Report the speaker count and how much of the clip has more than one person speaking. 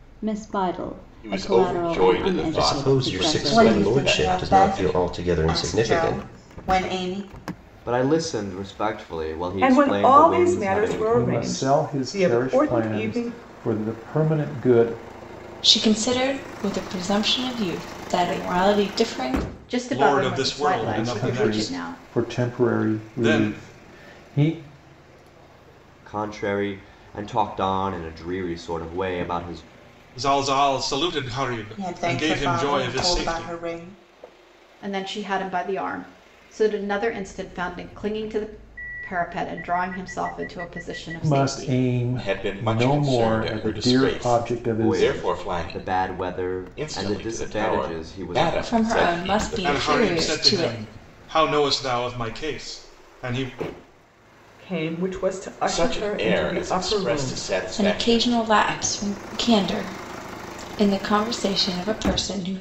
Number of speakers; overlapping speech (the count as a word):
ten, about 43%